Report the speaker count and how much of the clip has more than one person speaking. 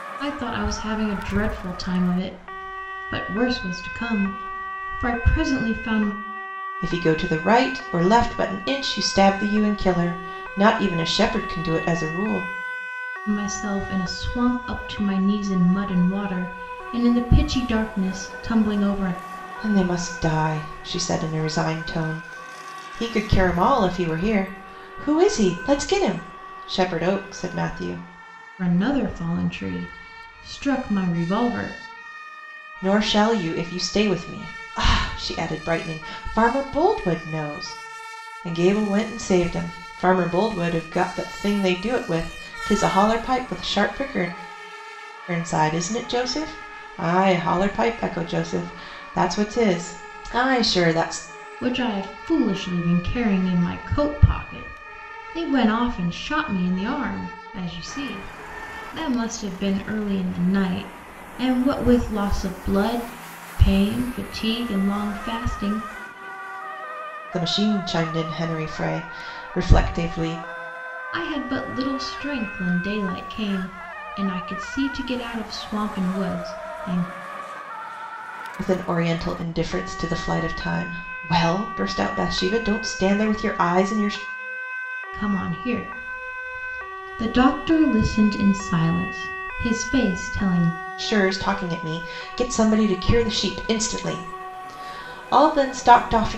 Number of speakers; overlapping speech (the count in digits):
2, no overlap